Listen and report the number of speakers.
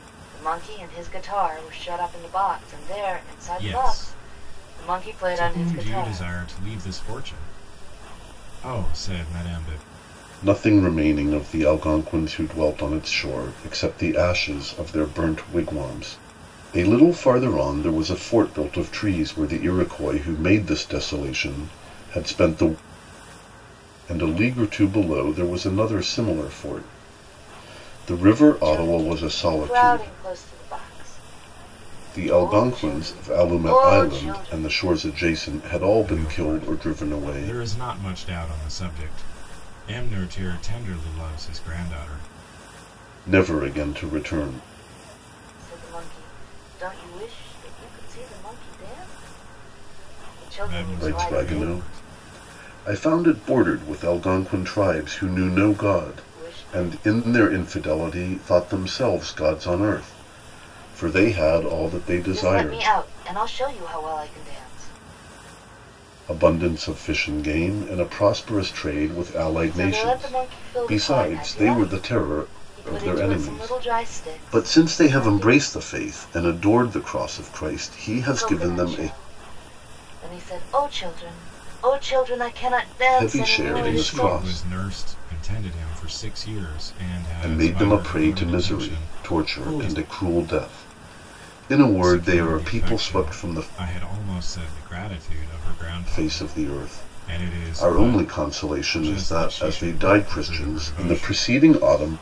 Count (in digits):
3